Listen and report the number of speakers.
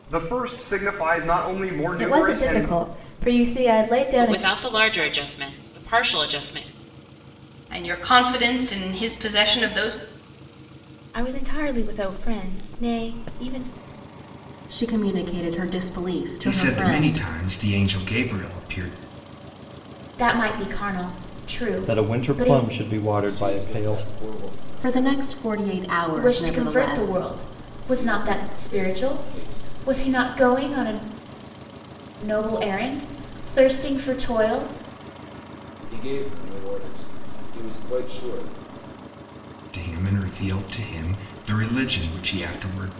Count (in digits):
10